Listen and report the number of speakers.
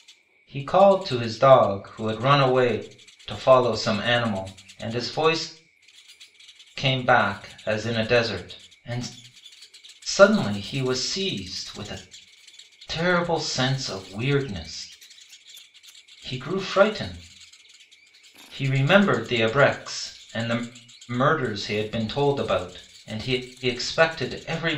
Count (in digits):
1